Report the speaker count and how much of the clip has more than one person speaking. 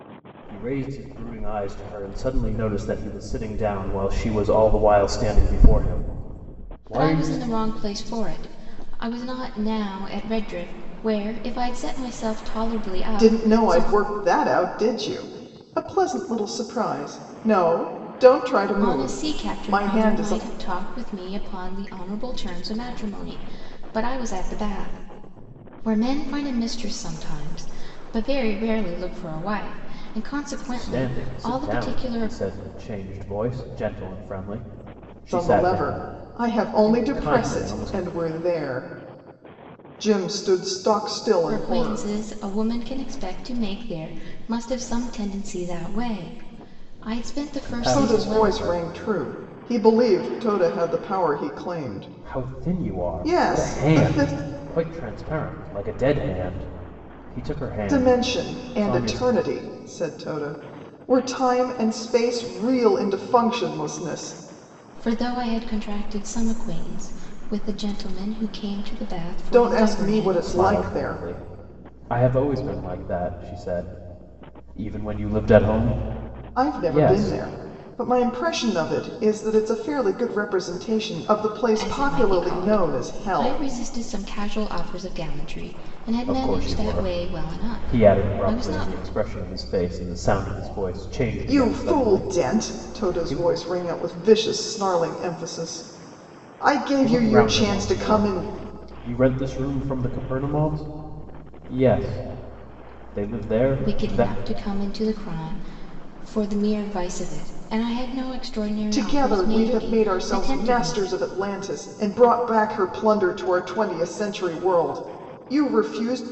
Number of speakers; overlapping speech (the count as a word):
three, about 22%